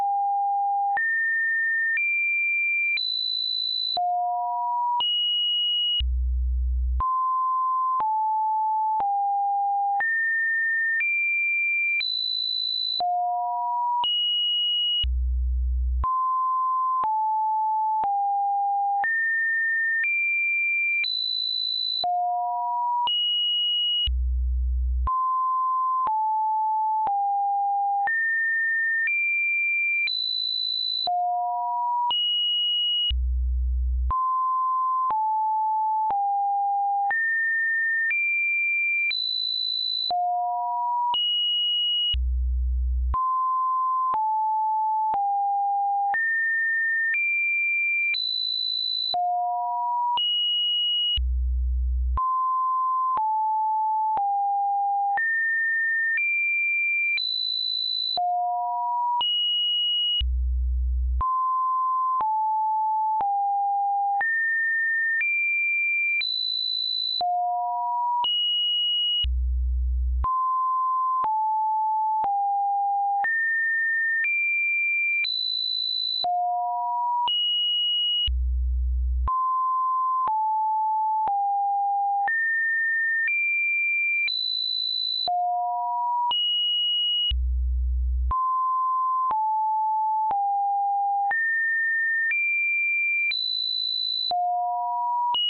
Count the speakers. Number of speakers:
0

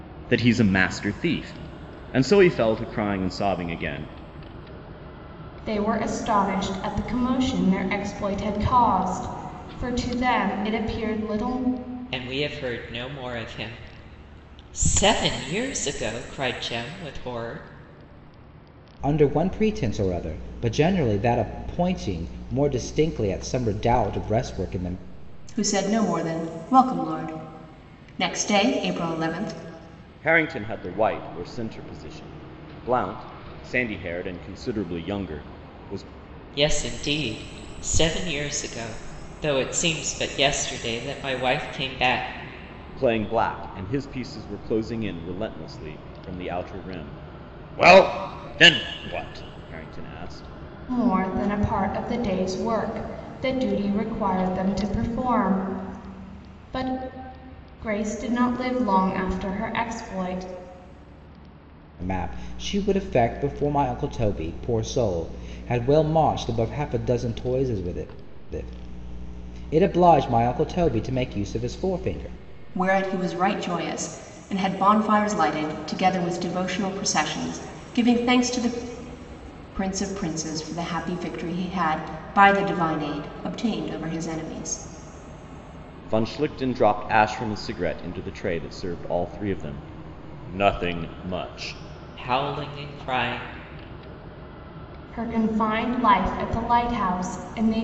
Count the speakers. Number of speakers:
5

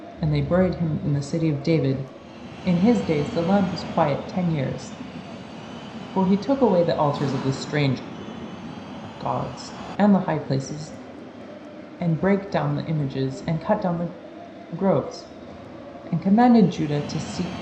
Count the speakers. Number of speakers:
1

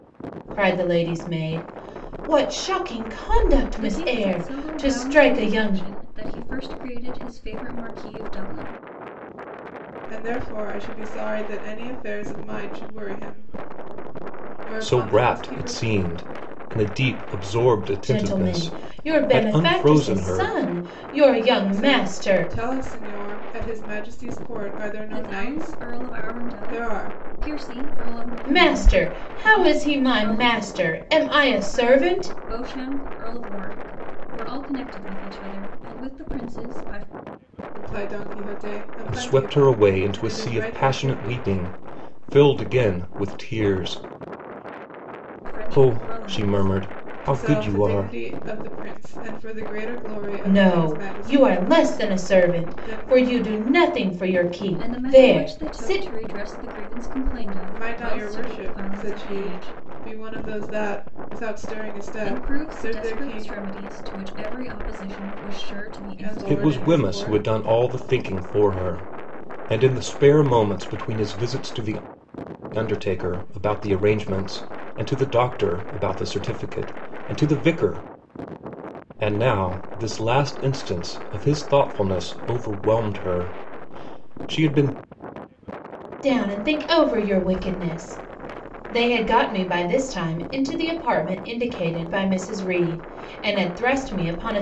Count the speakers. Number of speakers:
4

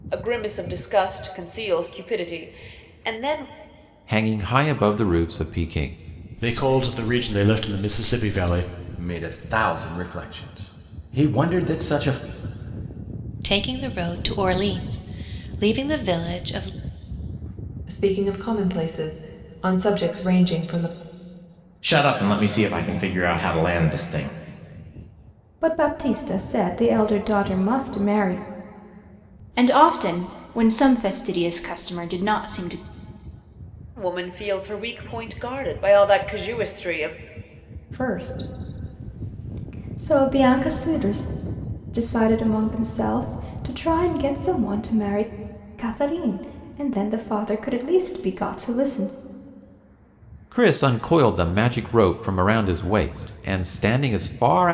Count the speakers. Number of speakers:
9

